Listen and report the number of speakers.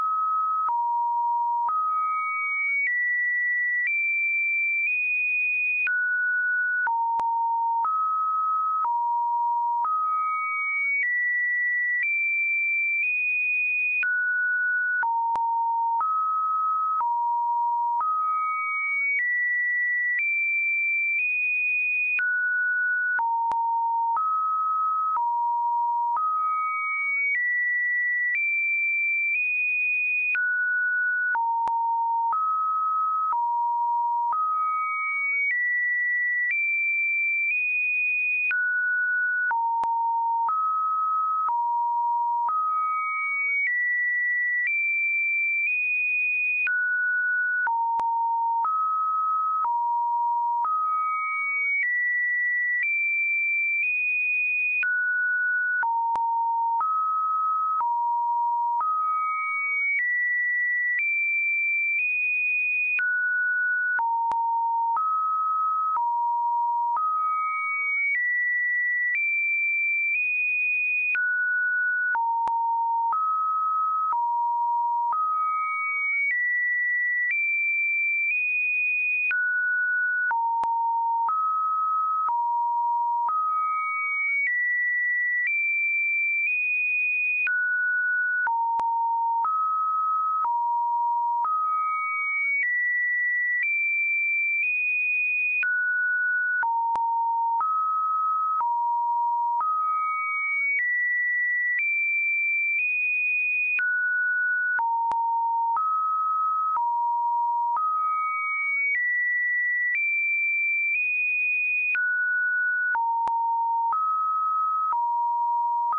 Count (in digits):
0